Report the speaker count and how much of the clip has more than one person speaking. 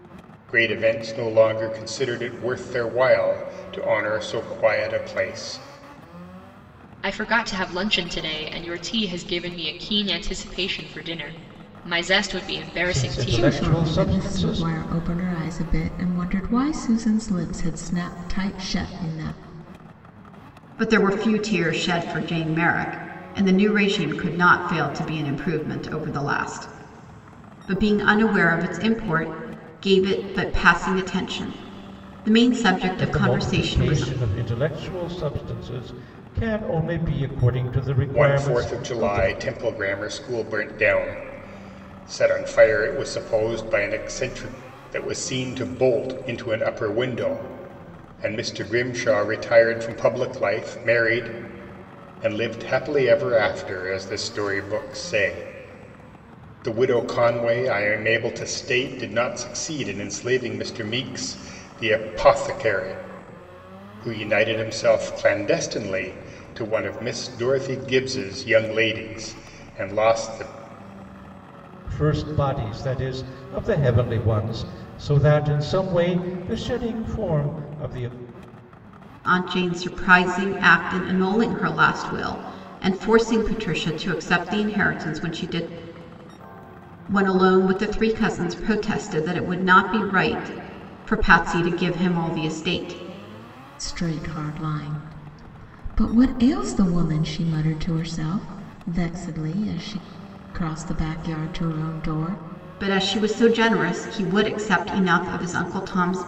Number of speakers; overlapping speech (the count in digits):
5, about 4%